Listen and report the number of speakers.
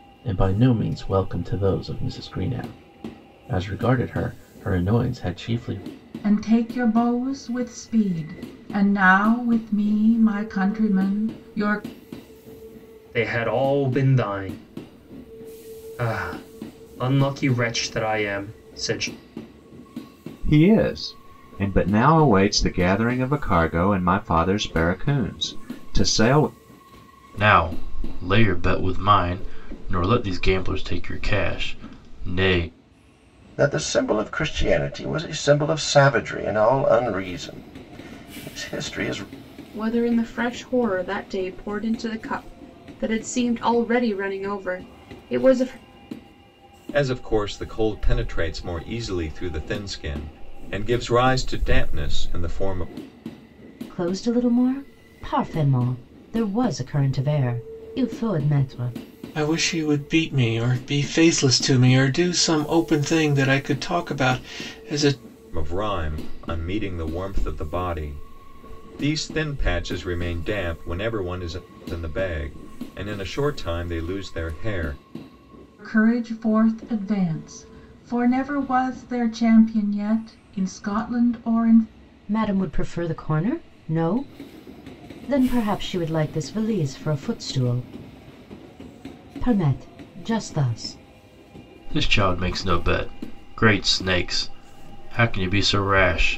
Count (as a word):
ten